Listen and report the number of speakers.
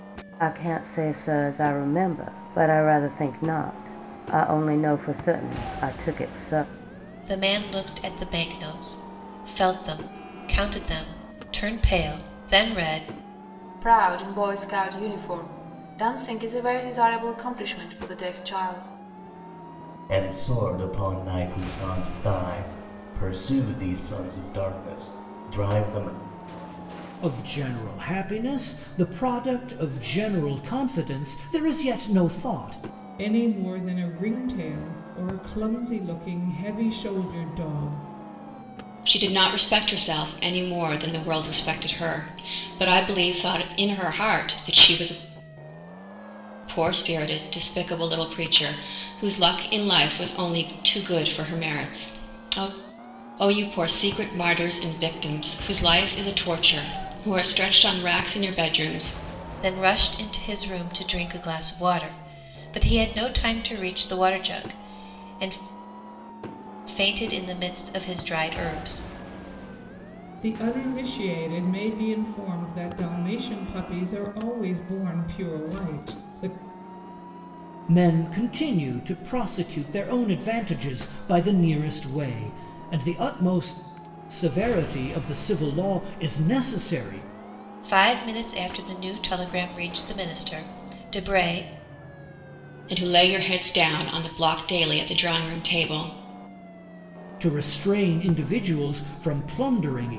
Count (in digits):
7